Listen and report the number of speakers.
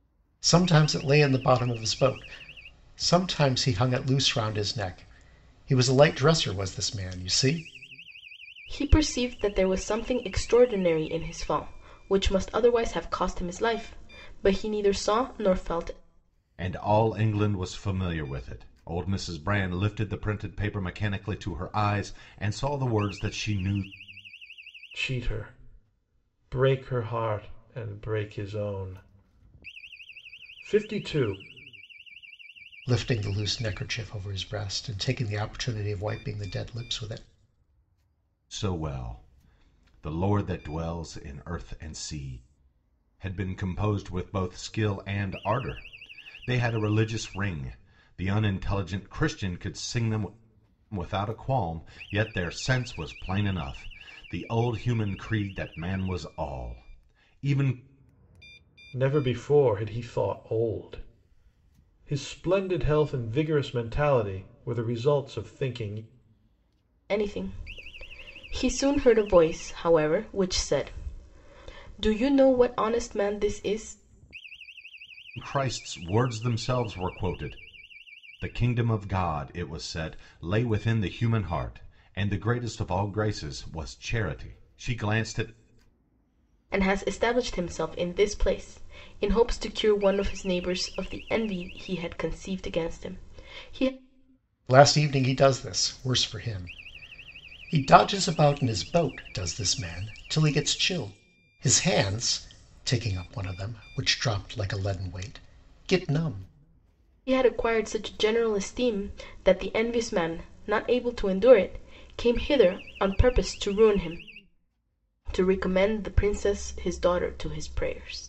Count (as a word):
four